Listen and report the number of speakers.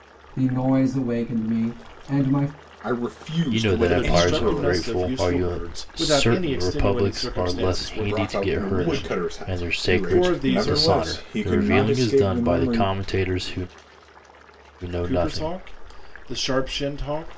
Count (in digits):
4